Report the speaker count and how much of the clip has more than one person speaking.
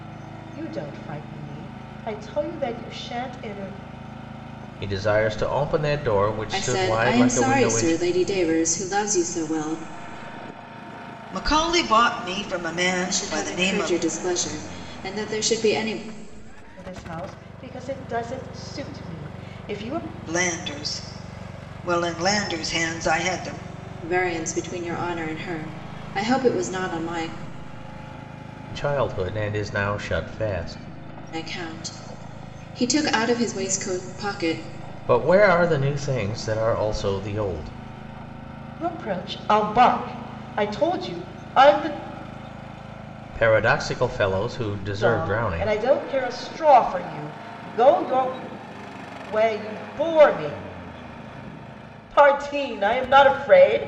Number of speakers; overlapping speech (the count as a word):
four, about 6%